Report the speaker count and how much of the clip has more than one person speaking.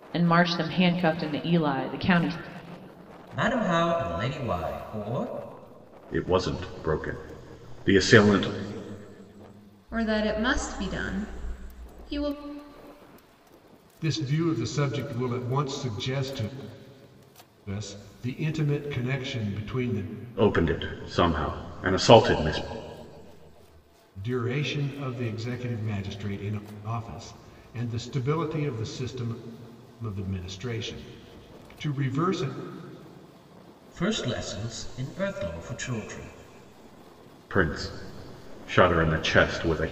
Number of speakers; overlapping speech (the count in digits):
5, no overlap